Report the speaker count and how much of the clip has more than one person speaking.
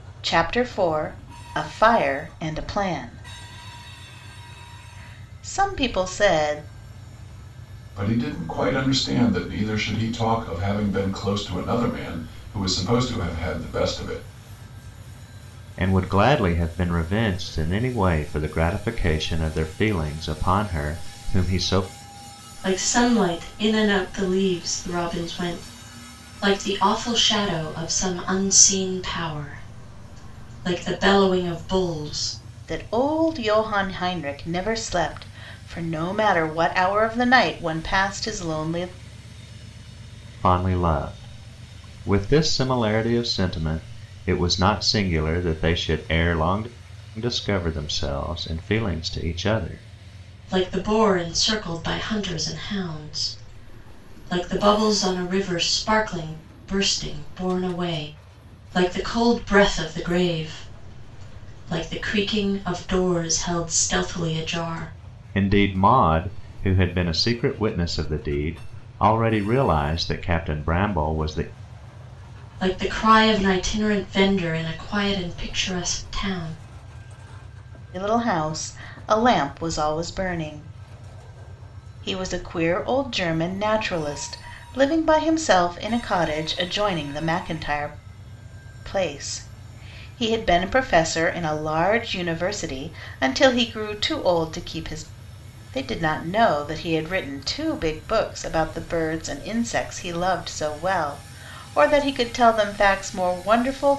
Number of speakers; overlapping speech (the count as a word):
four, no overlap